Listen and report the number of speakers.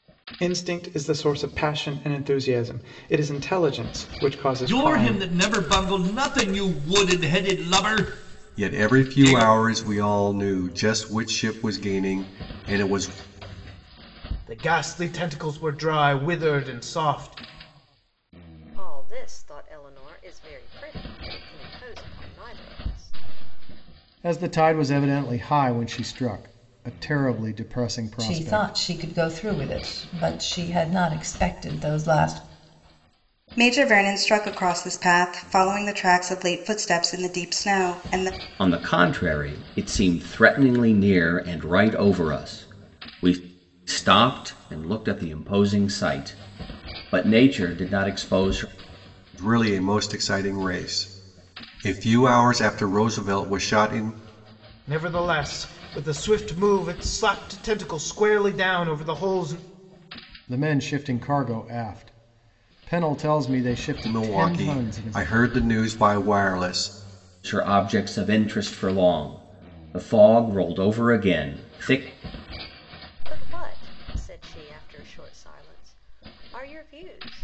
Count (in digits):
9